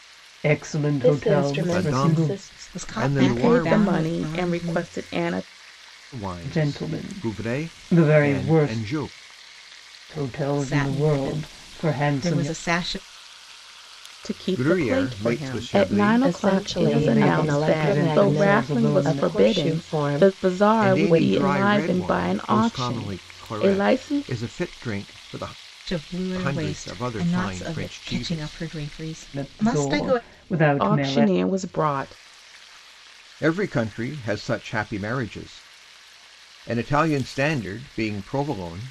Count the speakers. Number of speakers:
five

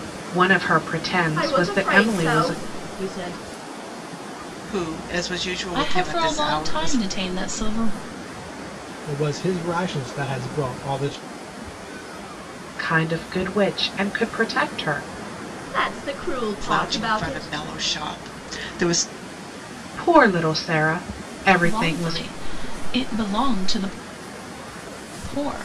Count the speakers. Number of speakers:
five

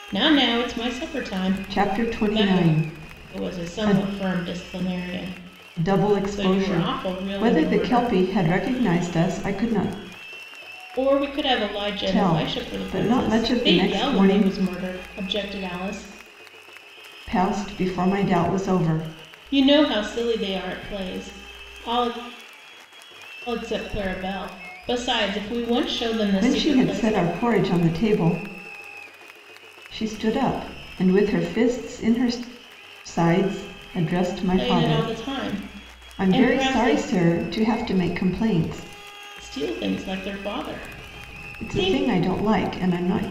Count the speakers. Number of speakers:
two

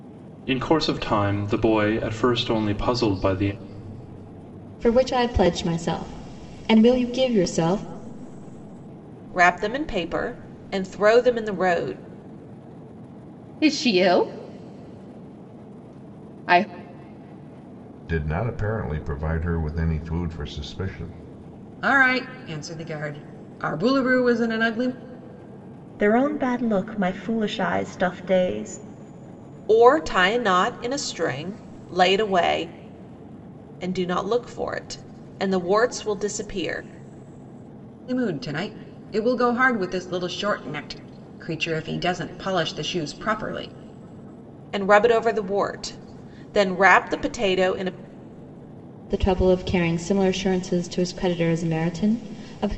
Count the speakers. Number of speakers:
seven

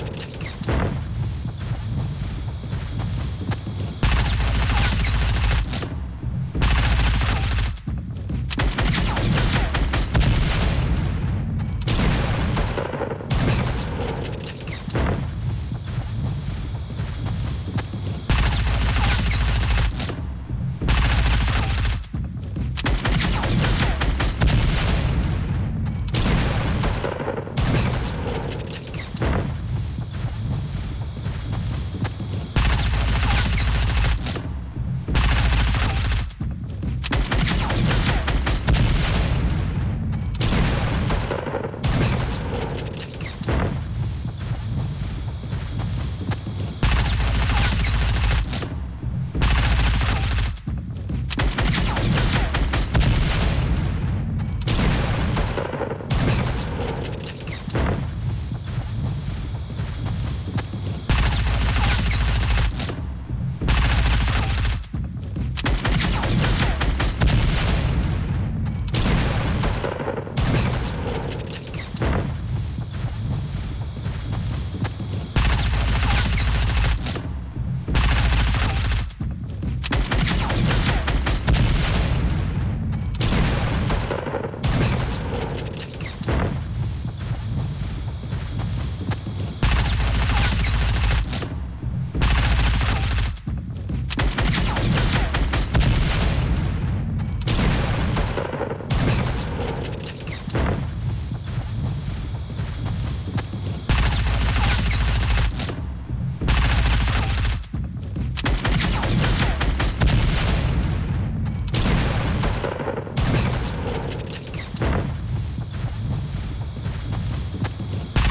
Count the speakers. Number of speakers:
zero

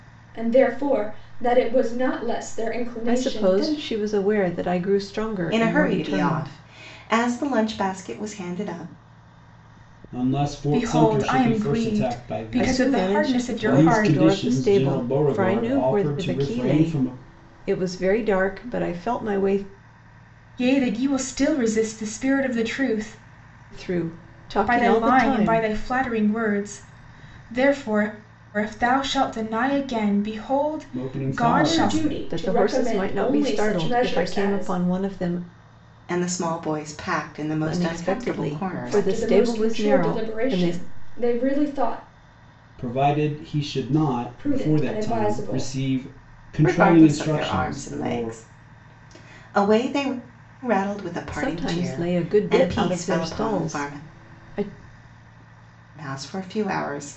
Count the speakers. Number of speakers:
five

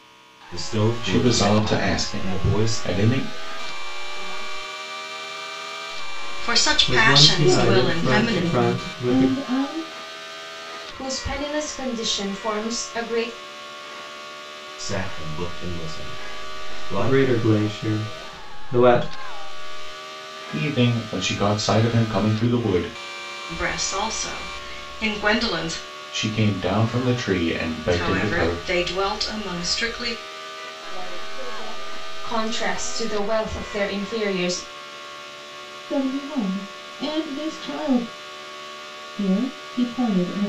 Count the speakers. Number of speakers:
eight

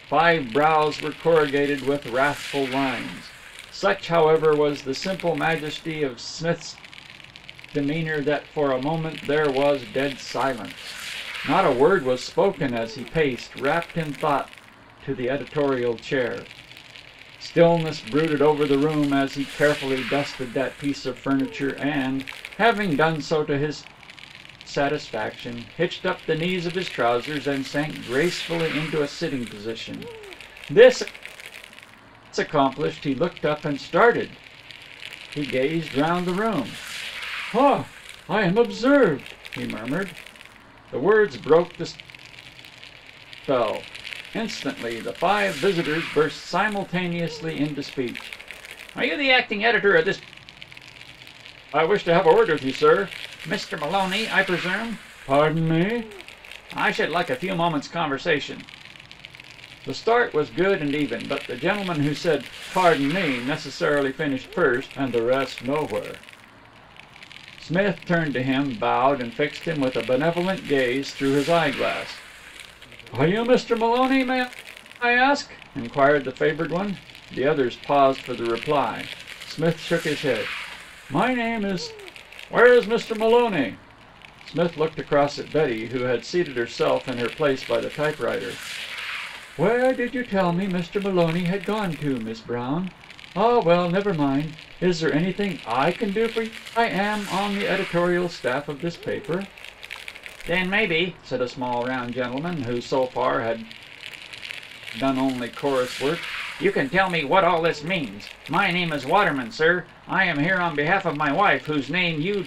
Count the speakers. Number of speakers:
one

